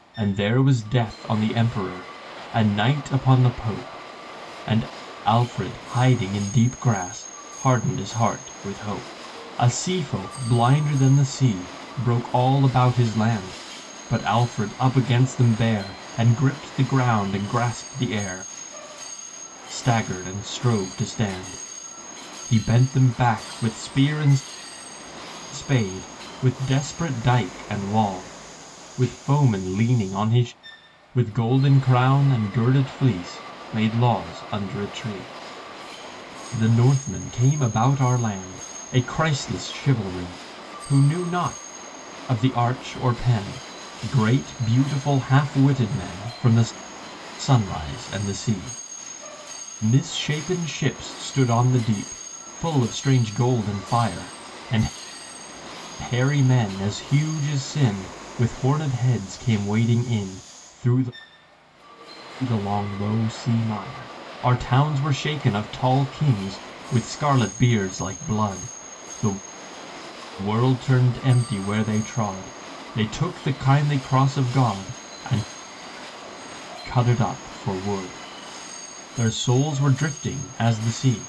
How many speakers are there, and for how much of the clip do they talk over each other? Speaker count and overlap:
1, no overlap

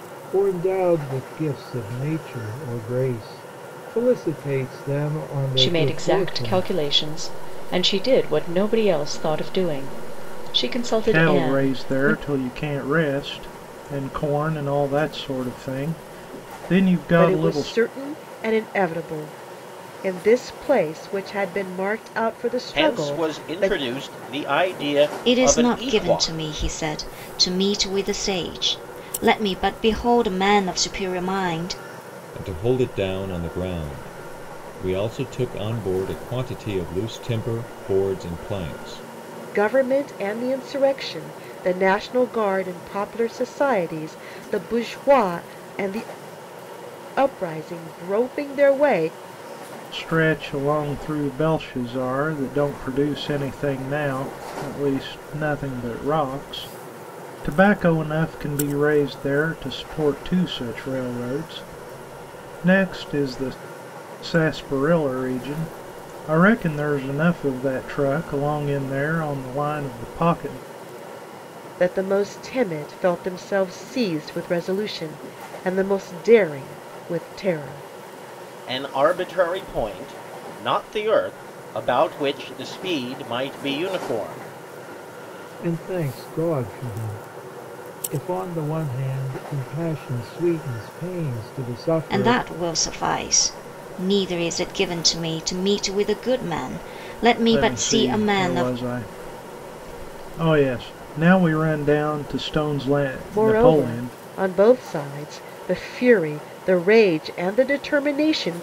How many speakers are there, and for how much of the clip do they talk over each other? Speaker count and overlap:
7, about 7%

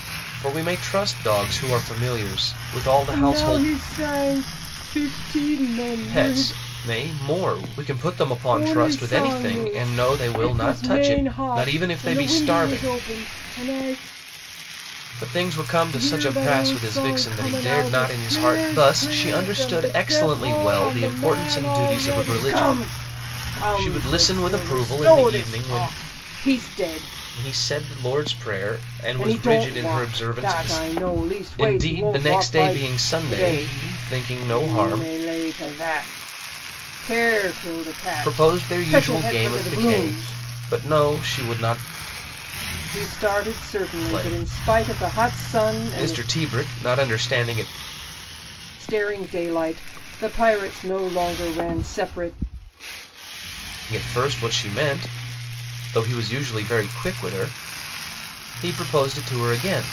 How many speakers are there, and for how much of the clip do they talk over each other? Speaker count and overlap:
2, about 40%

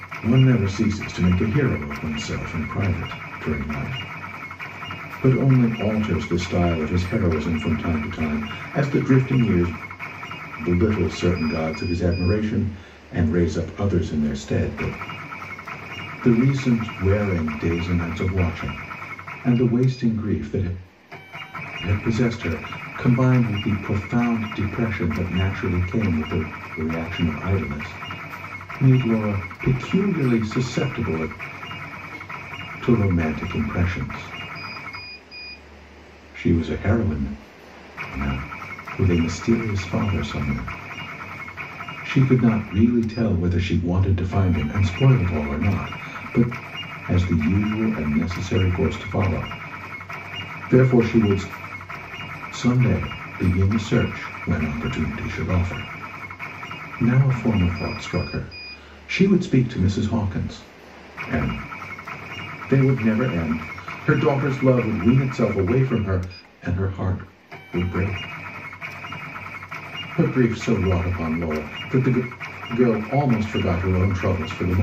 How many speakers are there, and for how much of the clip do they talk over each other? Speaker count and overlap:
1, no overlap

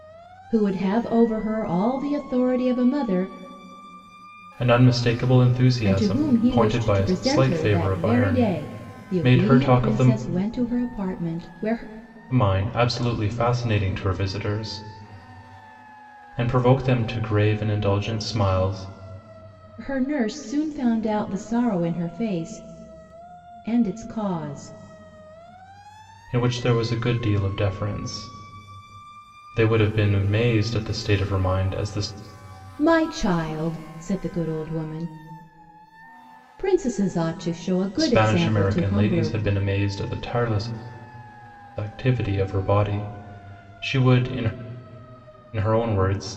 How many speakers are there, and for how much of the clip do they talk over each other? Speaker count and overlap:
2, about 12%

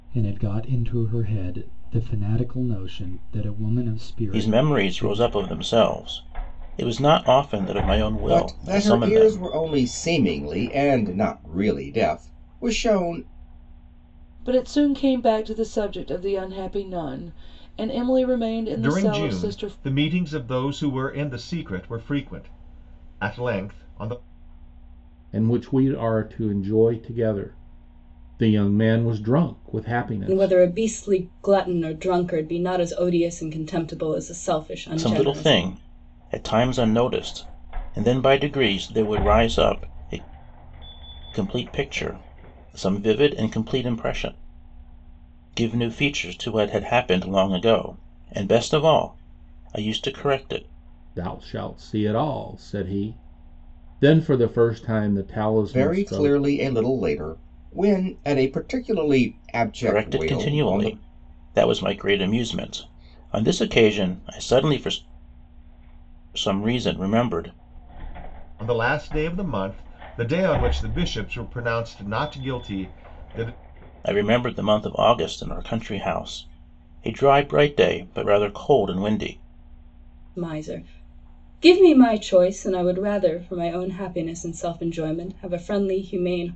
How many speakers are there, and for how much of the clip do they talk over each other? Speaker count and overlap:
7, about 7%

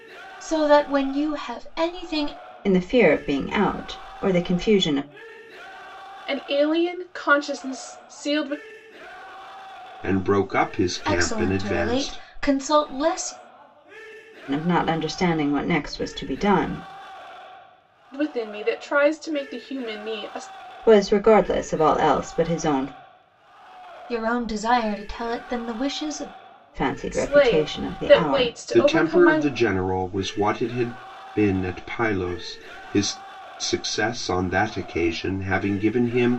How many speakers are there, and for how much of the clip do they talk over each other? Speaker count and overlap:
4, about 9%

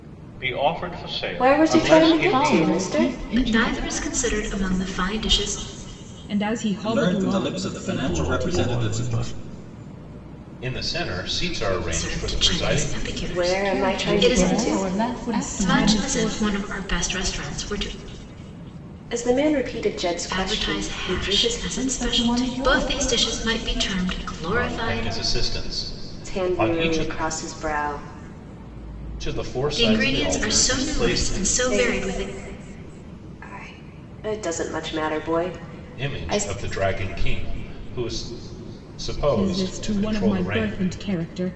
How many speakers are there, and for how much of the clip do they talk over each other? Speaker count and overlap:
8, about 43%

